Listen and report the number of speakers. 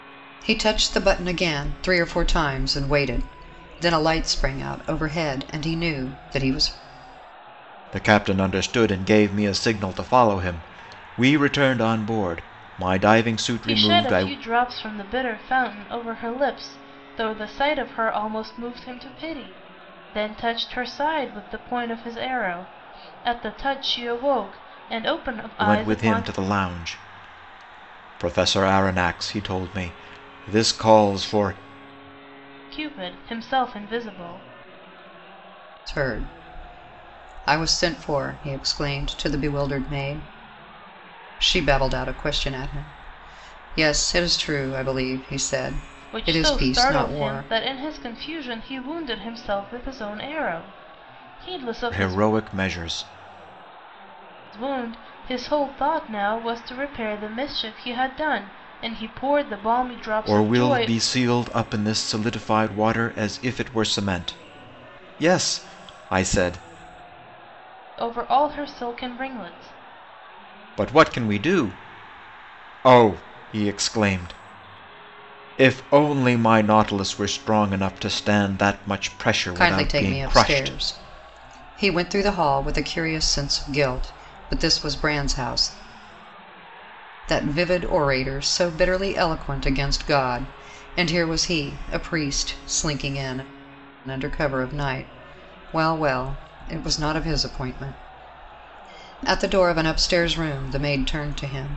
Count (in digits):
3